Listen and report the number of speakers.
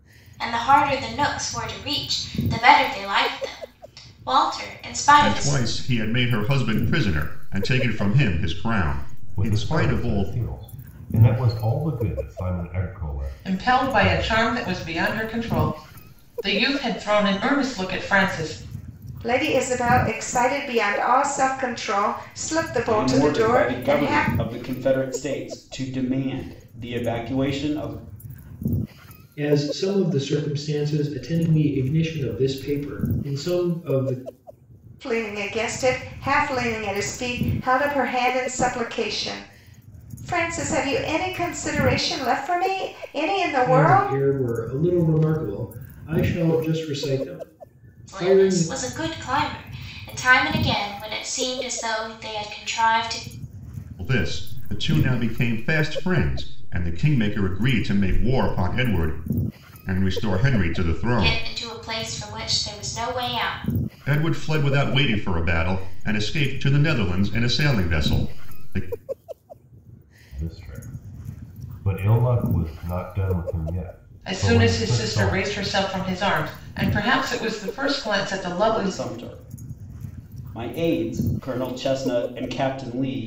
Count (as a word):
seven